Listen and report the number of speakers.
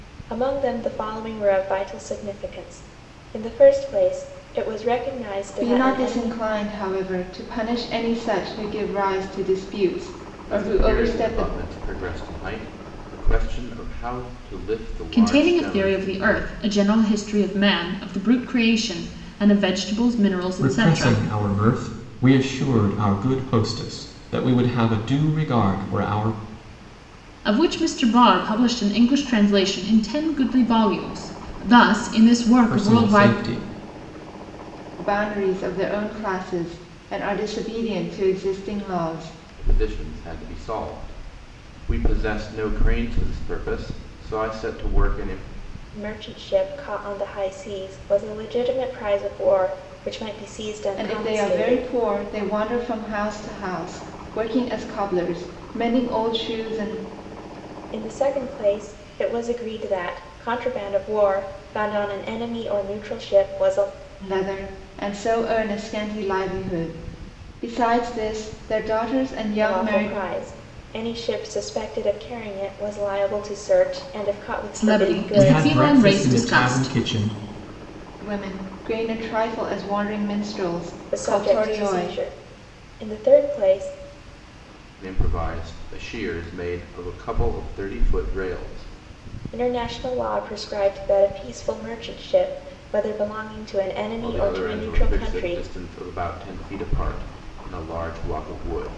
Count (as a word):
five